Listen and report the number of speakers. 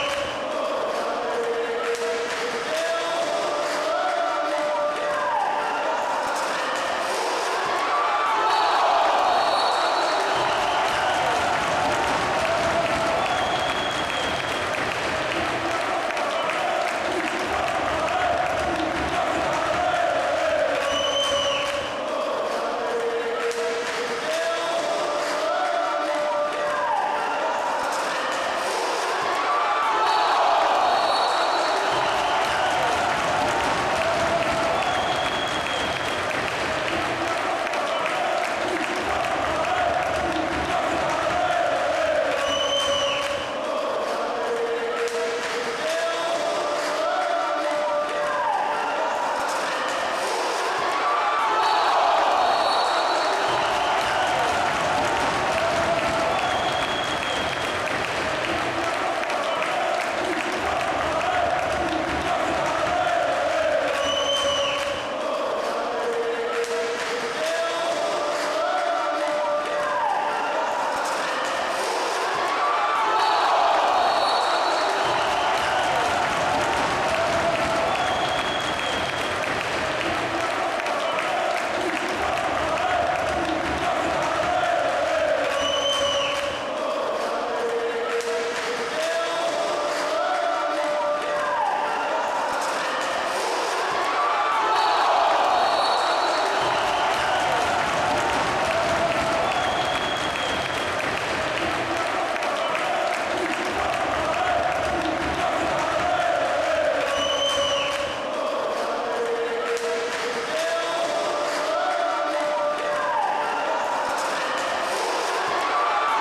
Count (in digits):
0